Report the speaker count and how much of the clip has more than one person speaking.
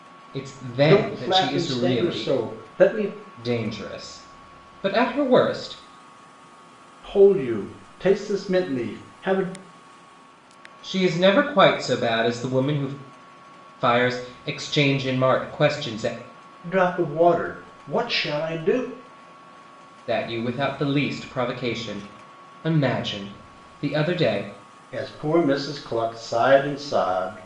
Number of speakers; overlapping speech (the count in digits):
2, about 5%